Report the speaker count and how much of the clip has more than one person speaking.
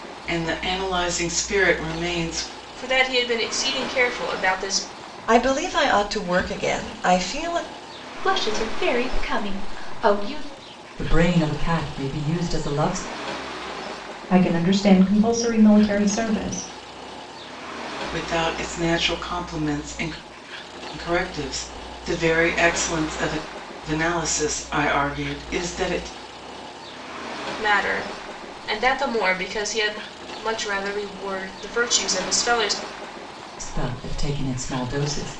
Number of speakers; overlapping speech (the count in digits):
6, no overlap